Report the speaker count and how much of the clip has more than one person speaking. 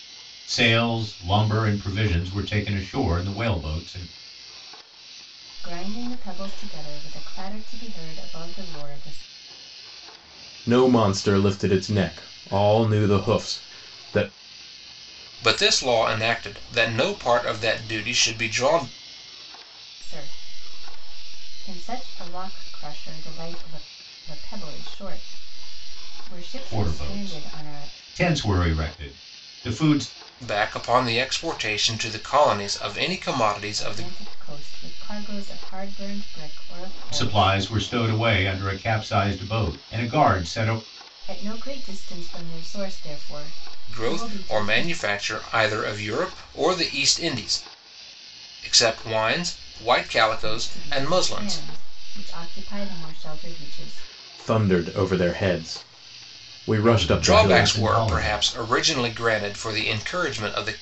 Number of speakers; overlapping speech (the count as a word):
four, about 10%